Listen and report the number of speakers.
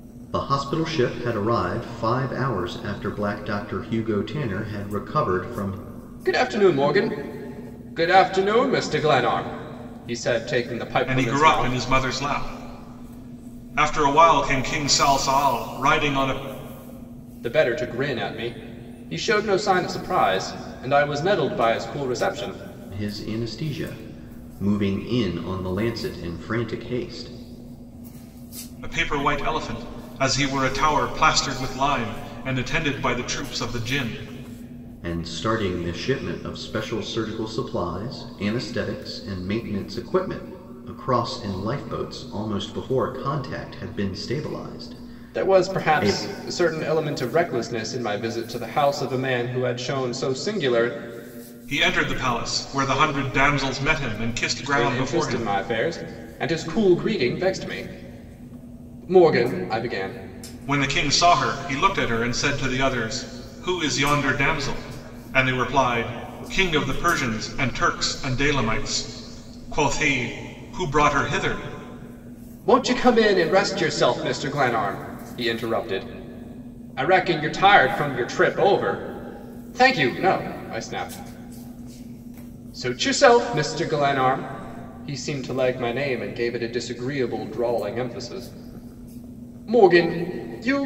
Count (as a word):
three